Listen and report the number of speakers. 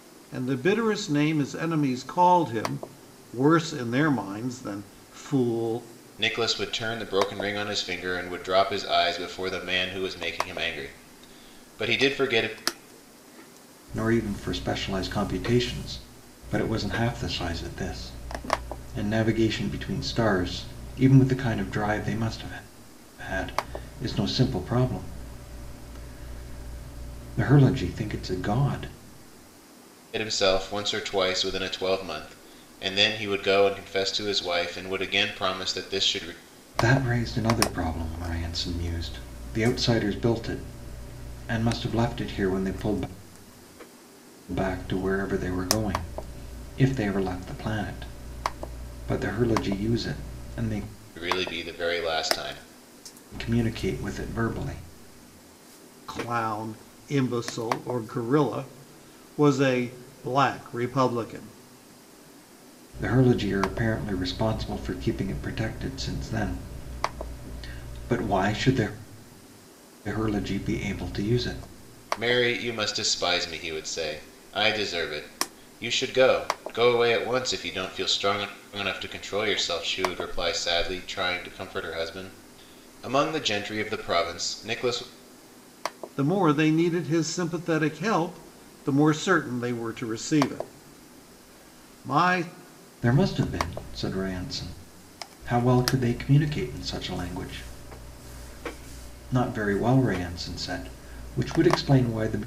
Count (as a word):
three